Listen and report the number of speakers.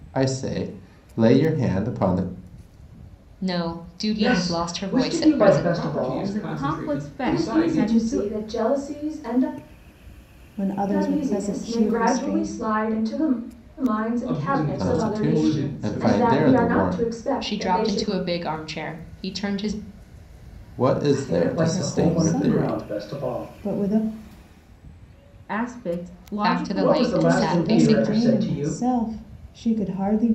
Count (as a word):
seven